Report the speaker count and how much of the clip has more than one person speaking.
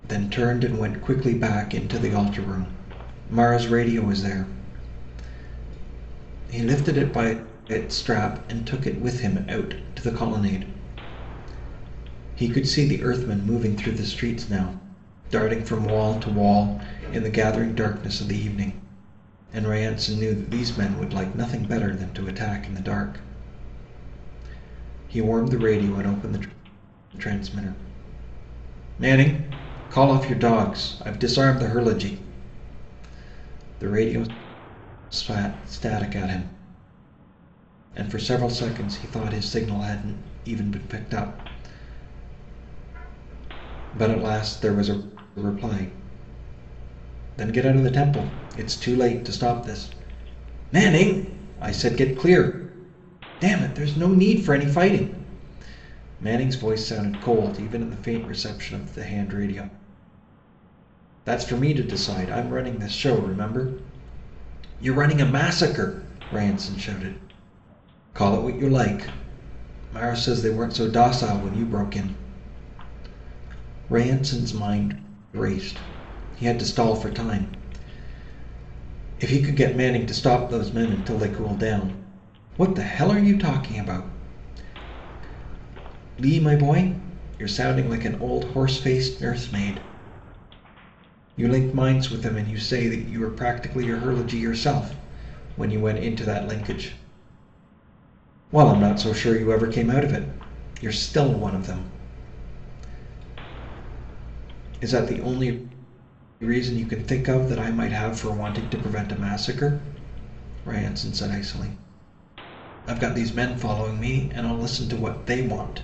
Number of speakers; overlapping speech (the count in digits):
1, no overlap